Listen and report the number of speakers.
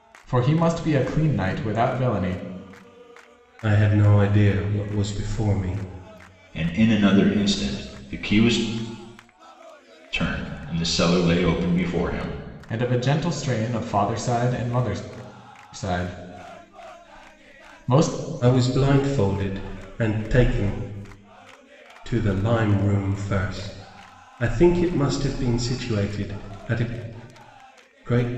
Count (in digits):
3